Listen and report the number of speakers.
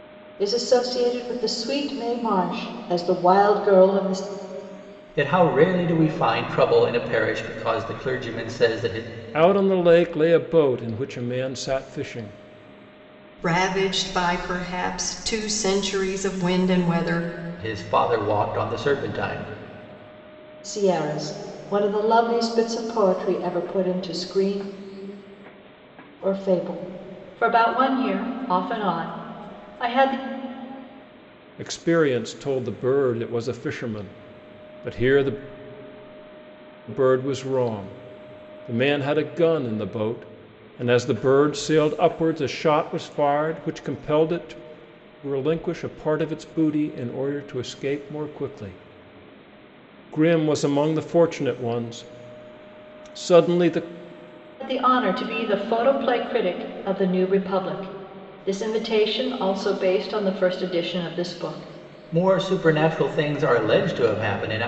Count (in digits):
4